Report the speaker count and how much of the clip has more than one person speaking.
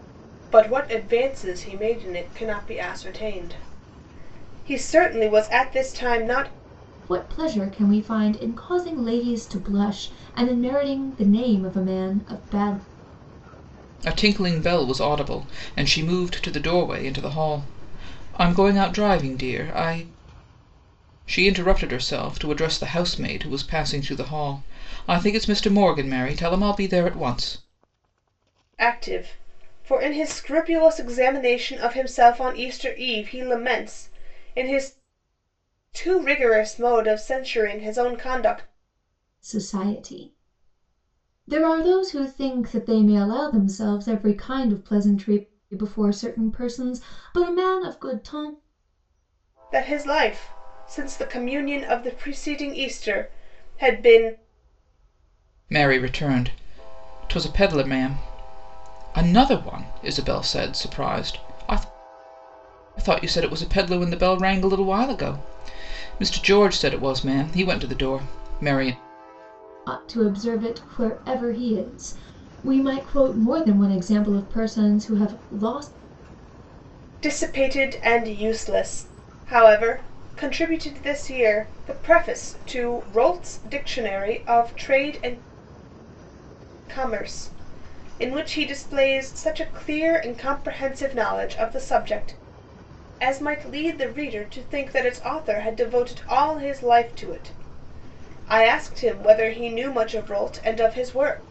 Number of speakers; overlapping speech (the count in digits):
3, no overlap